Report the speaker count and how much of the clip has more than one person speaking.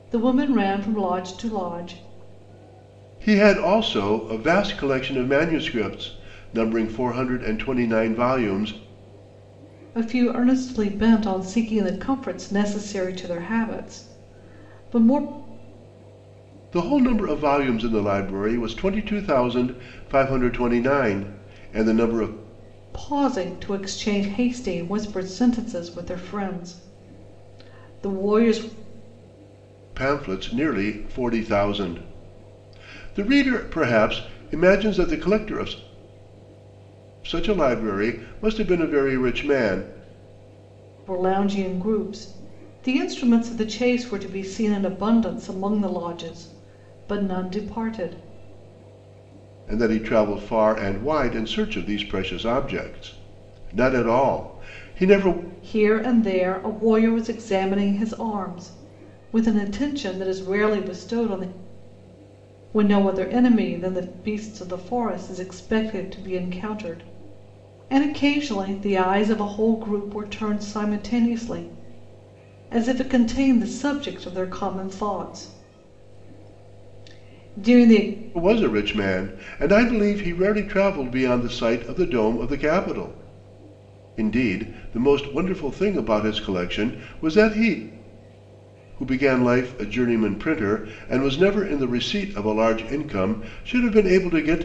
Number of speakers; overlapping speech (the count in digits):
2, no overlap